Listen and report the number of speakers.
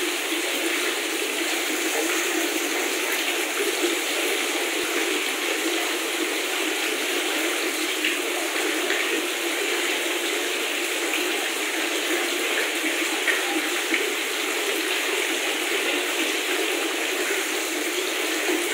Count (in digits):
0